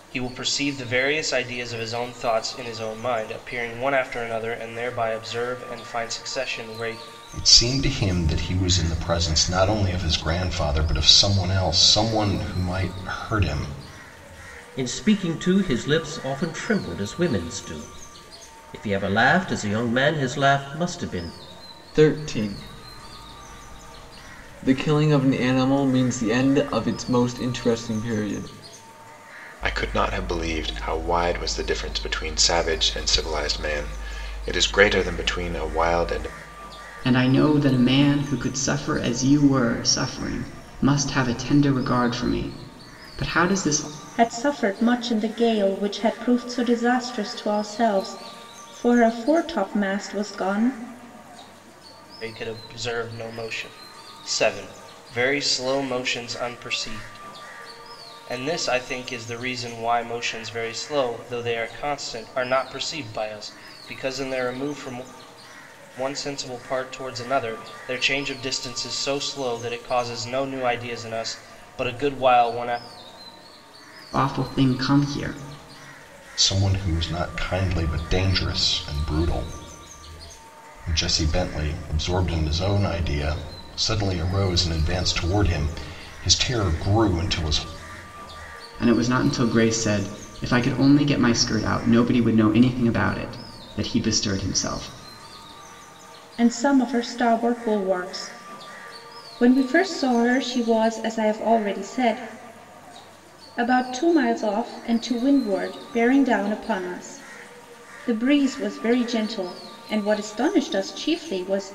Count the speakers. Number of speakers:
7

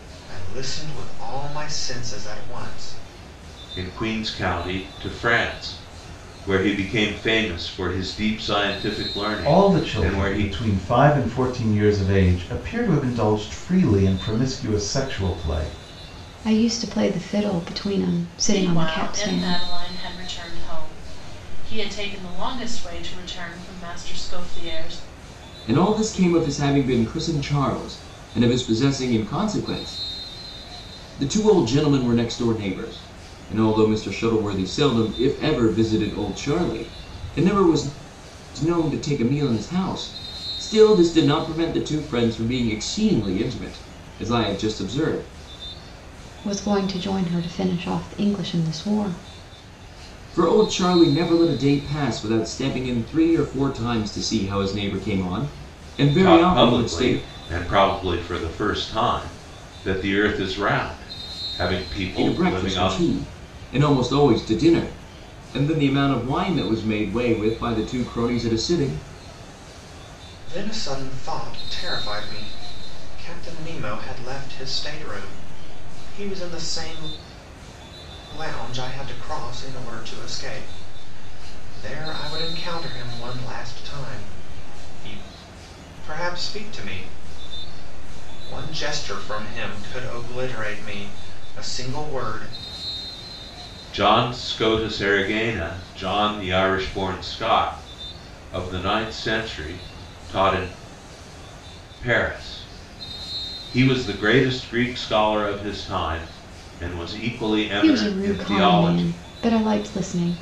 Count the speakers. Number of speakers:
6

